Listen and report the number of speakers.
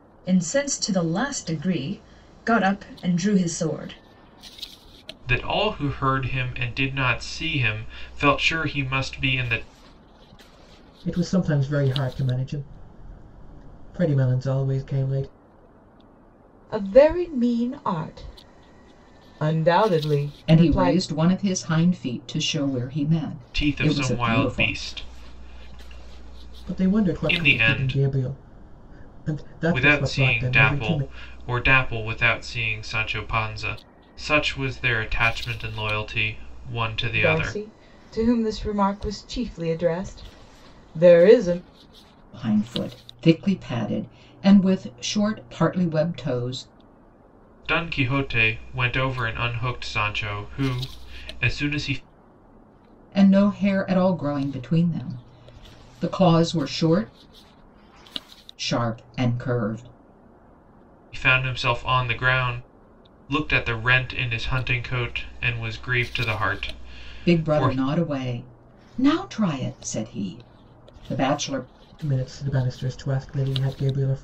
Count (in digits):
5